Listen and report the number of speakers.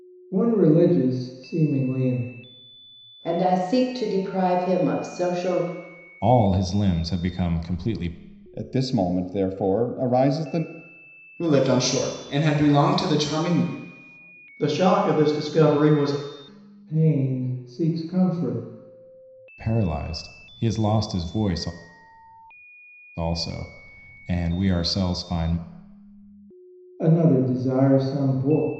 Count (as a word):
six